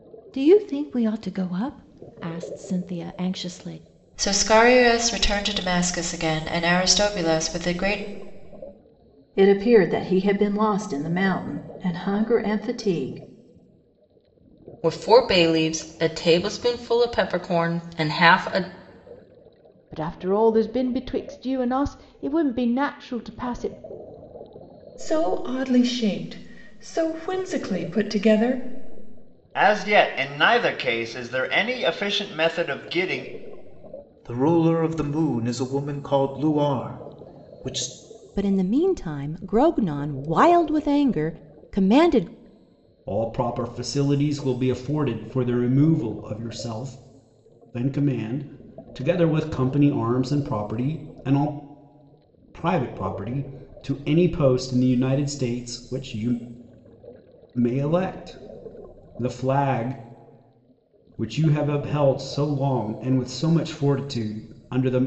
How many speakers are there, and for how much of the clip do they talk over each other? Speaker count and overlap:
ten, no overlap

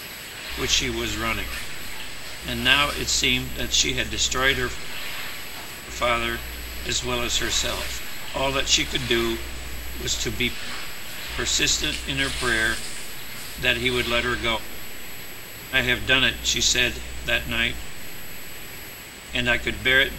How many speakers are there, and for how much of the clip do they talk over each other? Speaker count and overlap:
one, no overlap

